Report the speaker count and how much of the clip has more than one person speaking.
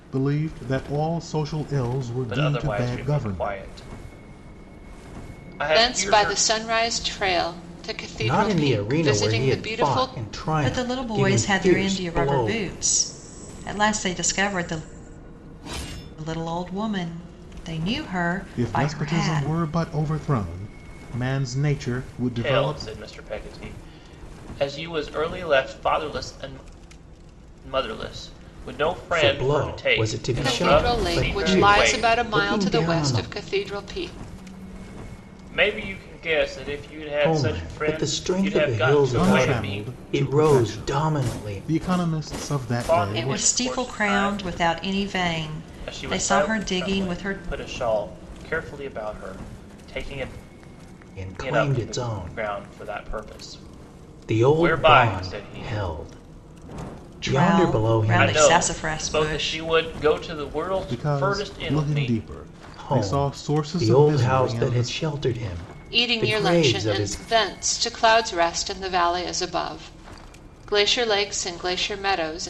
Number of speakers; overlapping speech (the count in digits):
5, about 41%